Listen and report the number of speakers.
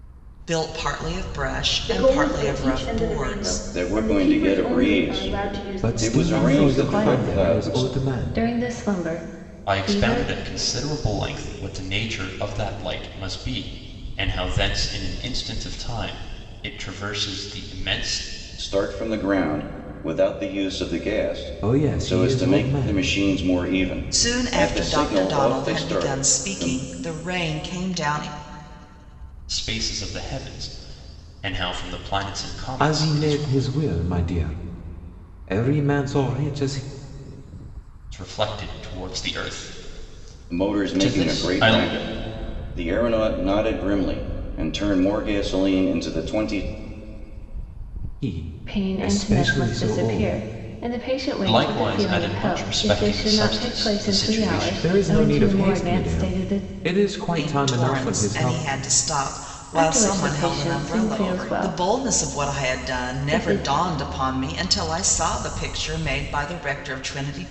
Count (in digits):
6